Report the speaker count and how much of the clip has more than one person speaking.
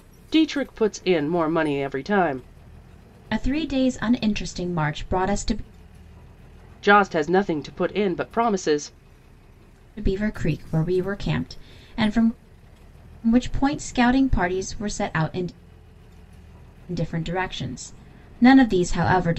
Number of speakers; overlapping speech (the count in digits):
2, no overlap